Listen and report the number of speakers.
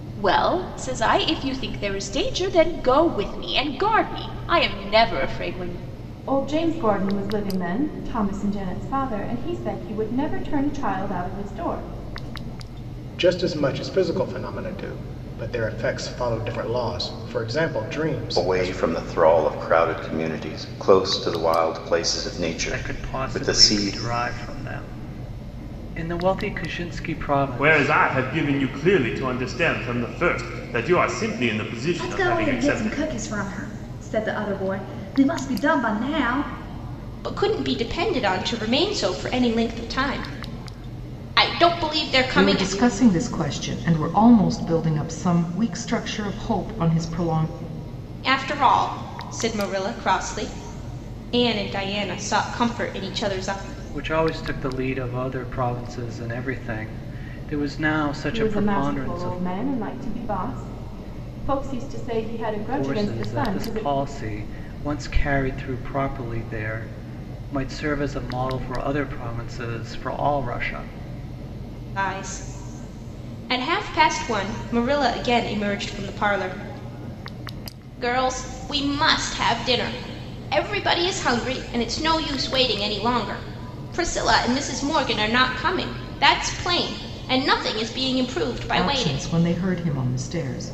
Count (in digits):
9